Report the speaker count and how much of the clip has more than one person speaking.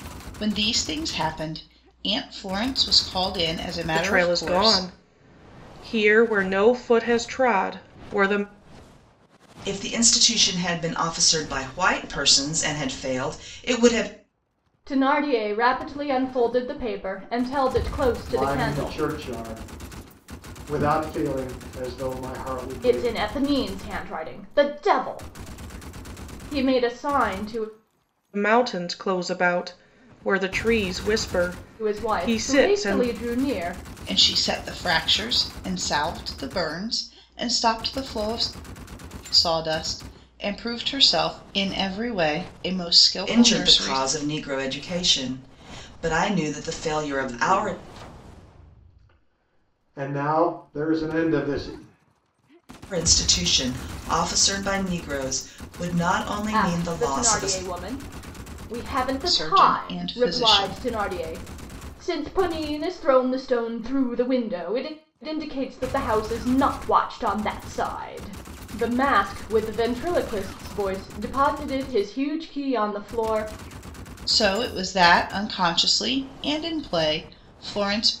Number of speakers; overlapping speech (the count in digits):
5, about 9%